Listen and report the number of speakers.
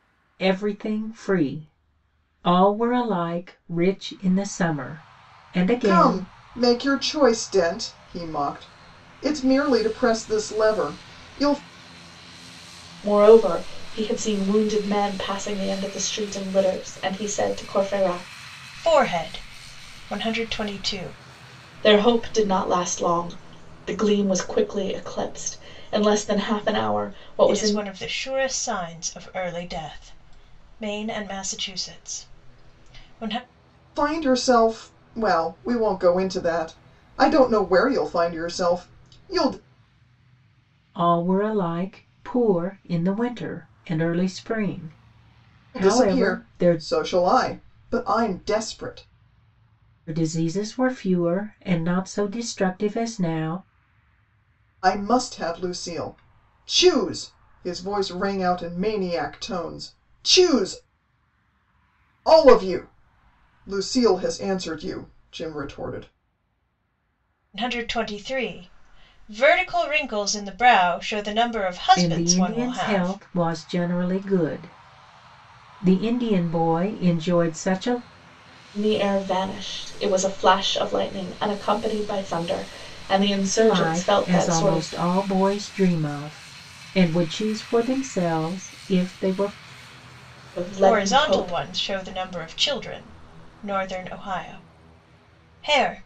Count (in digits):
4